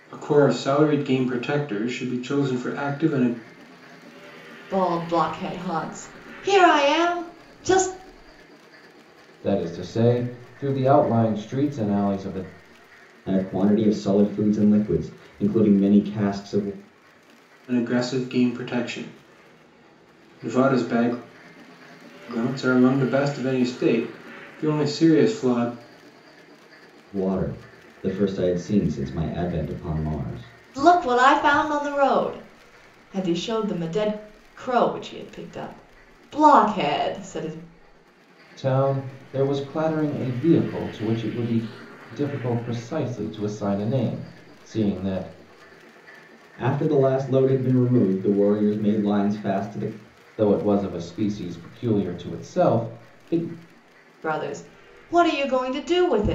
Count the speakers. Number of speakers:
4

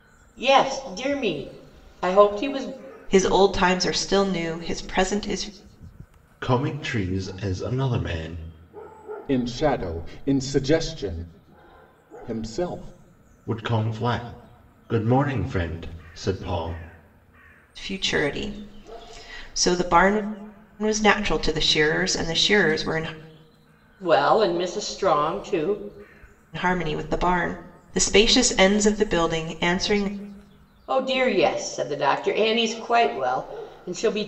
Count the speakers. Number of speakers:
4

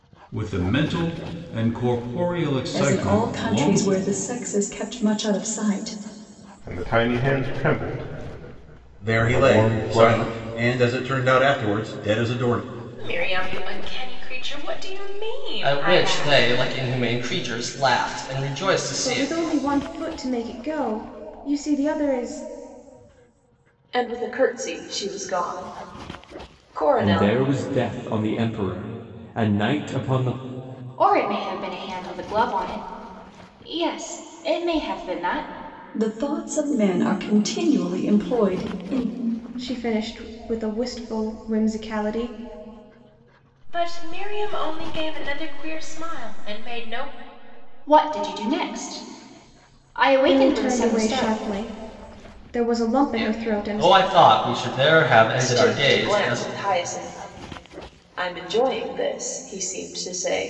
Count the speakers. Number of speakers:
10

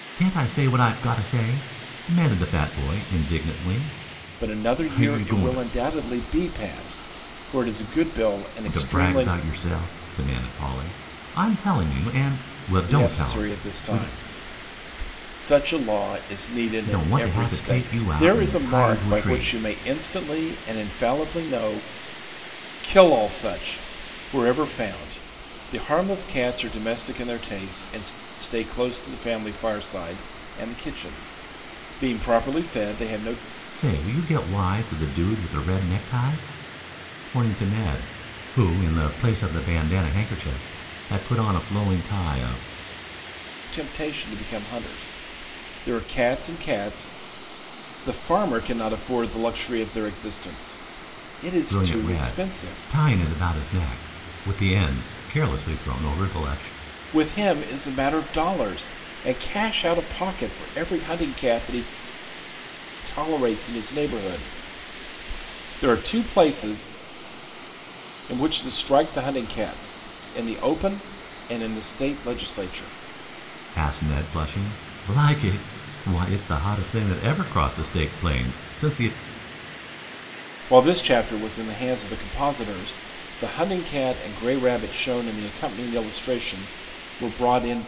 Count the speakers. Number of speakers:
2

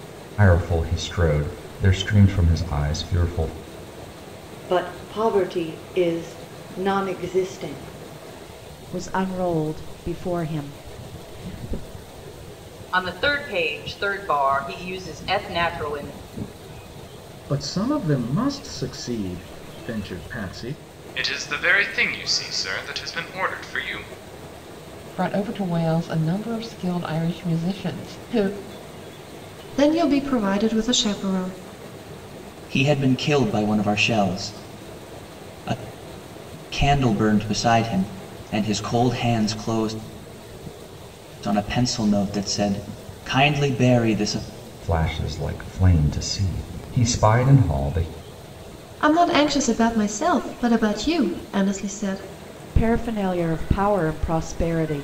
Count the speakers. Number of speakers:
9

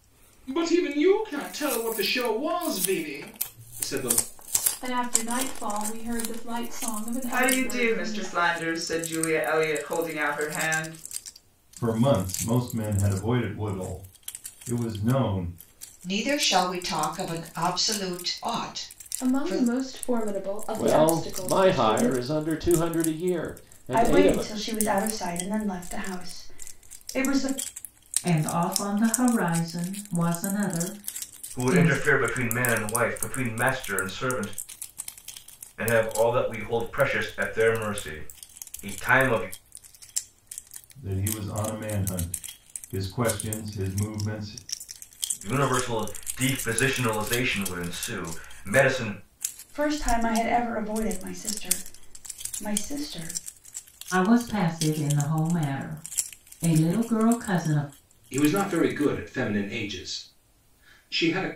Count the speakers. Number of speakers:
10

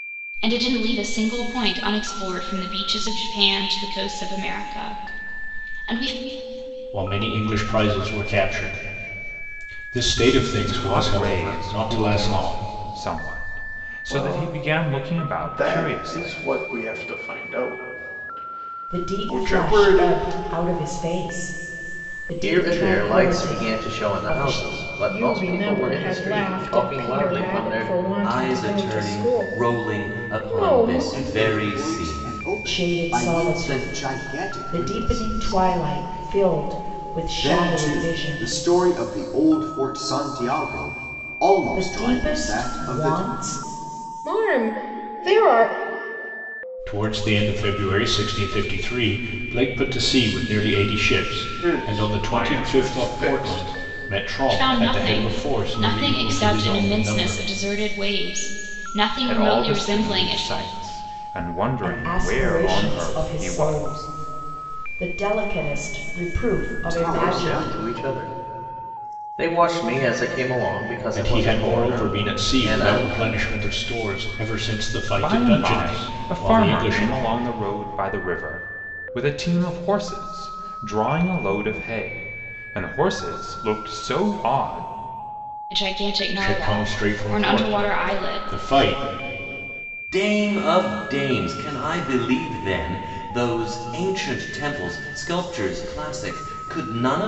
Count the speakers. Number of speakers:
9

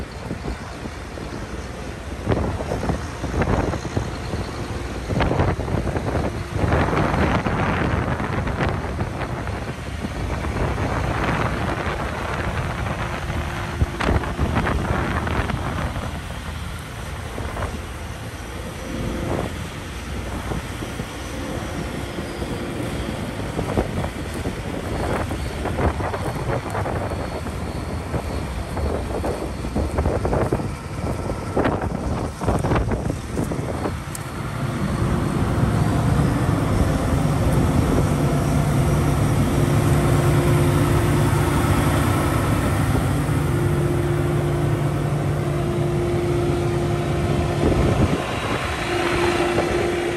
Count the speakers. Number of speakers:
0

